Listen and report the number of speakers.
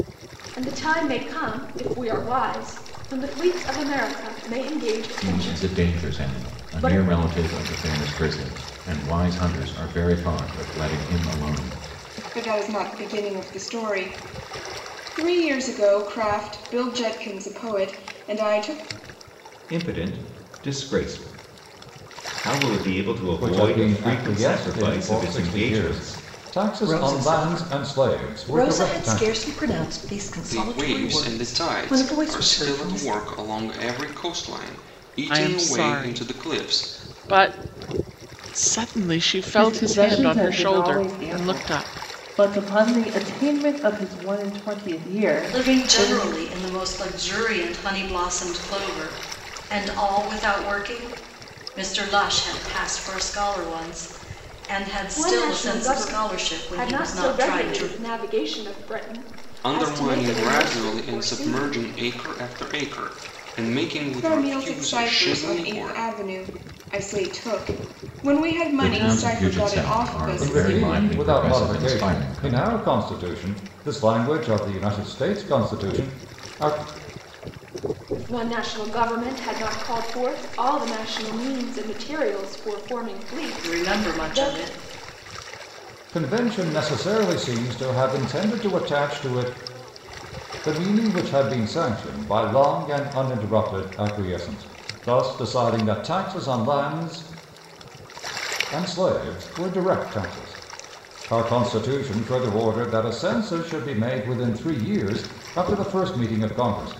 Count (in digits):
10